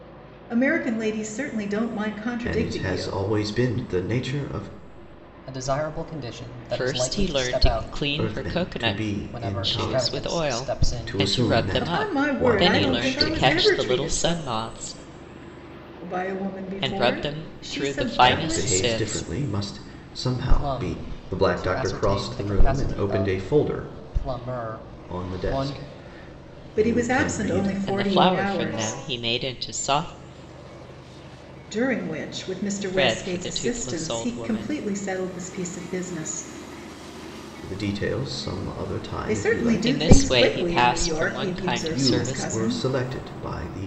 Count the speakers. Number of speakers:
four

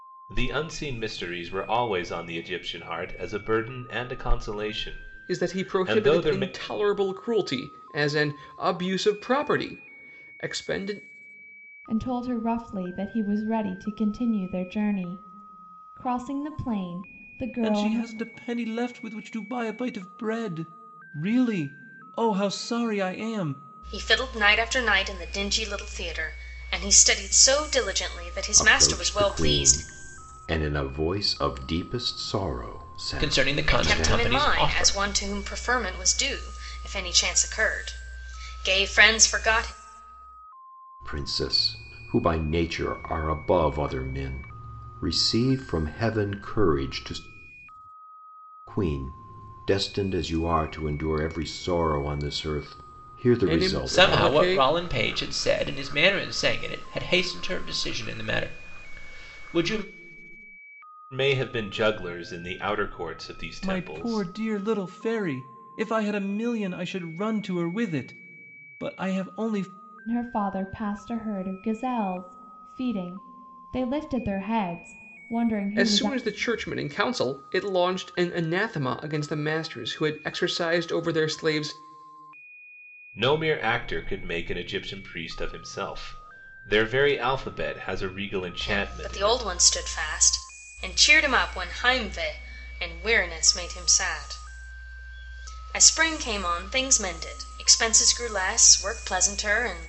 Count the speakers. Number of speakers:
seven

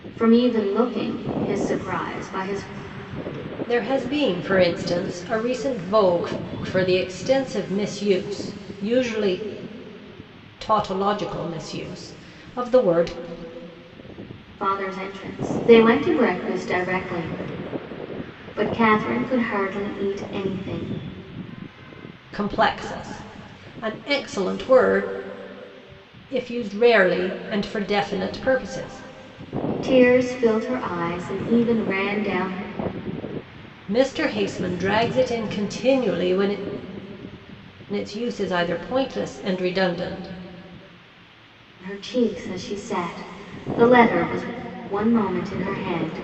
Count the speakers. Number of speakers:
two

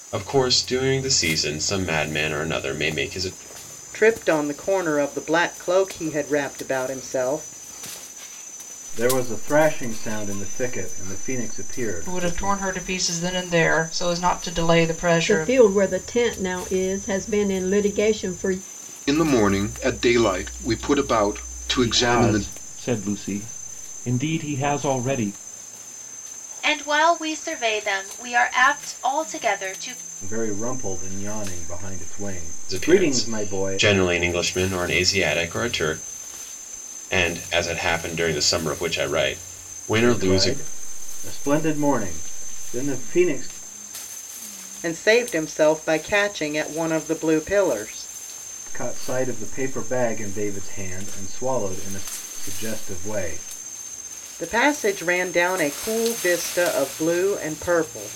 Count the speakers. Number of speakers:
eight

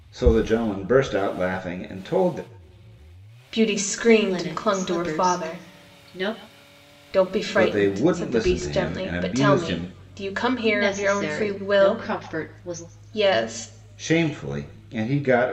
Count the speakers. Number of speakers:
three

